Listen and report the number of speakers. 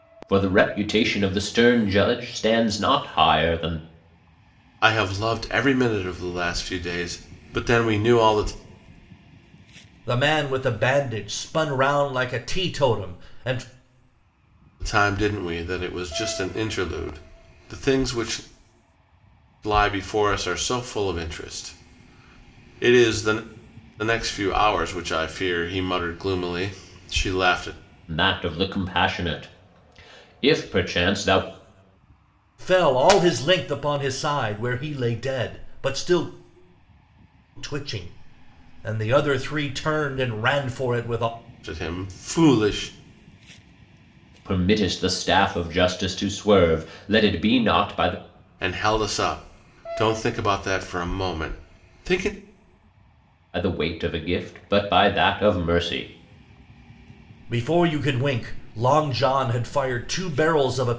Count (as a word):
three